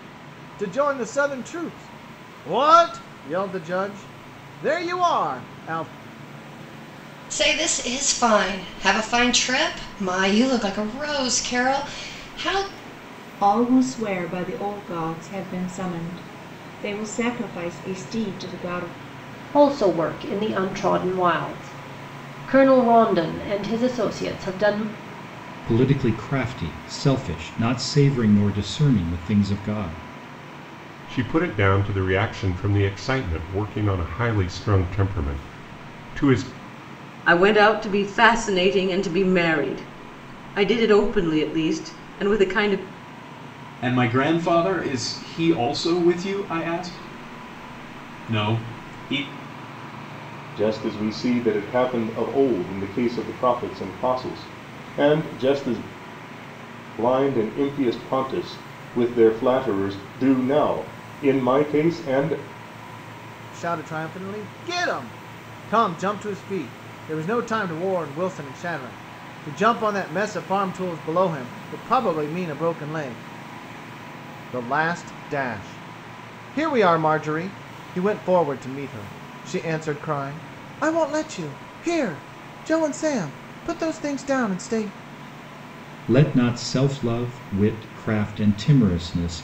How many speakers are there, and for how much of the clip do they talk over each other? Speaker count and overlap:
9, no overlap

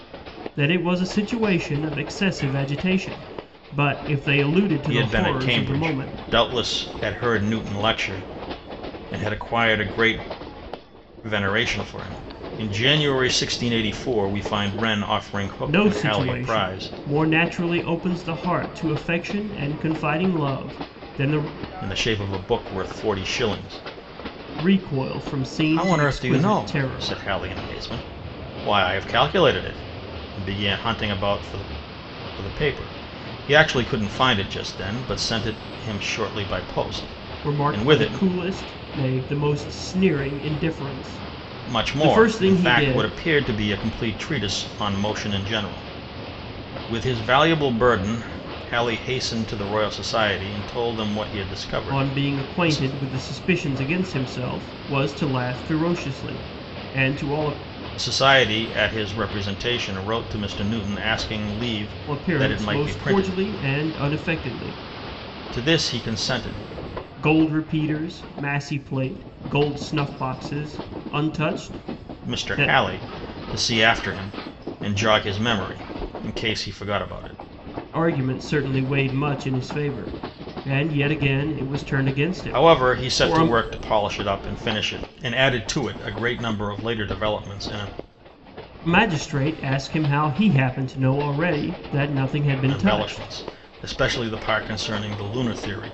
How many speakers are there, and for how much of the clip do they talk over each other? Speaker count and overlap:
2, about 12%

